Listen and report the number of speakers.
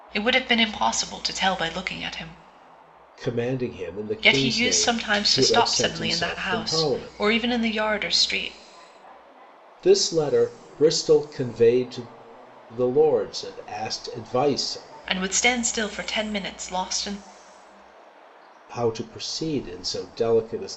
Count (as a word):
two